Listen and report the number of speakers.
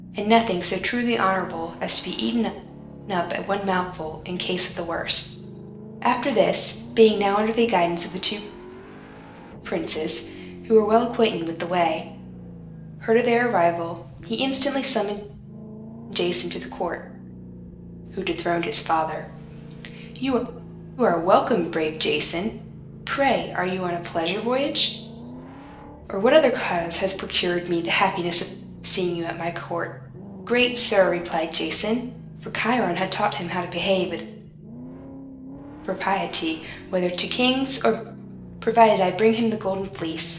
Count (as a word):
one